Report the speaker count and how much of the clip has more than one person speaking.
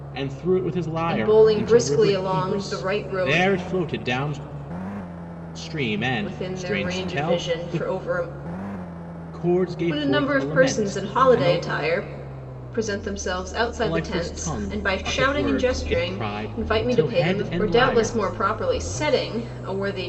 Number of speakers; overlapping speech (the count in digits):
2, about 51%